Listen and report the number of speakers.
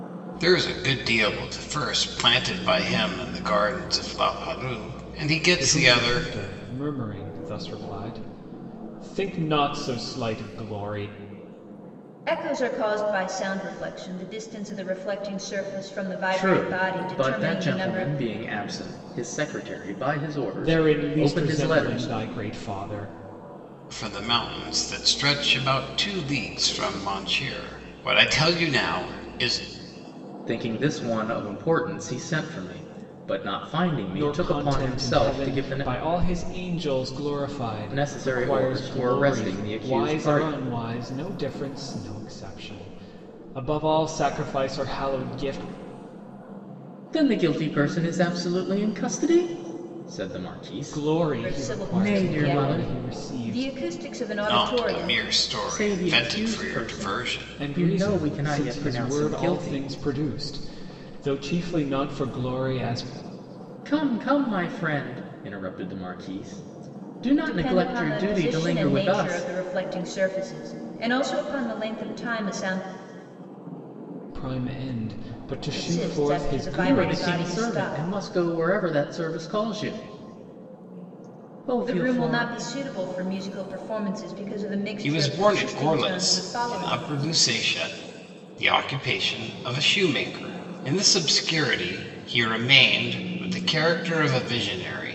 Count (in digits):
4